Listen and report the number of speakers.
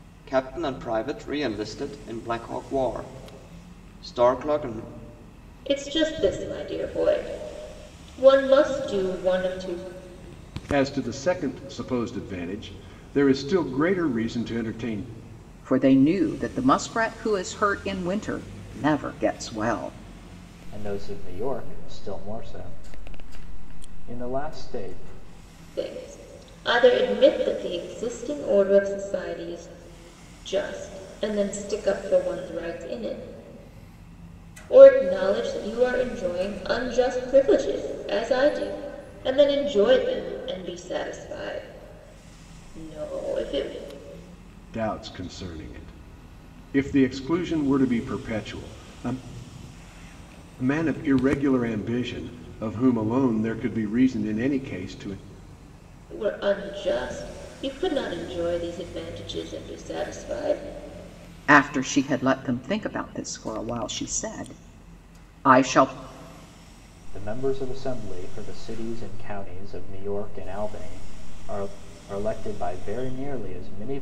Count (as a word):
five